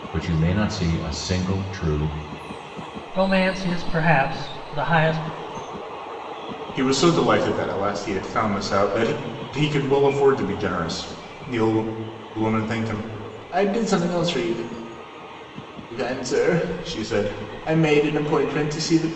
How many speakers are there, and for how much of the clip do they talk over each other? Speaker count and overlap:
three, no overlap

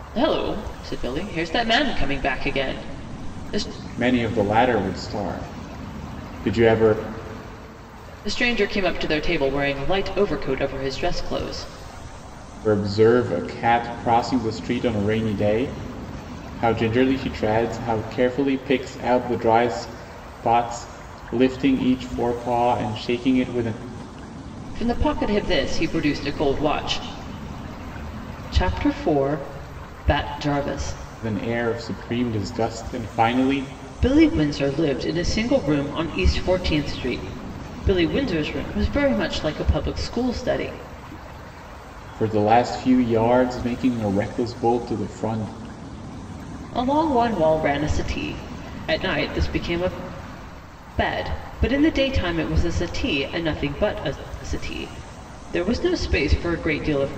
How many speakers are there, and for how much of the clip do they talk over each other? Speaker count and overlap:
two, no overlap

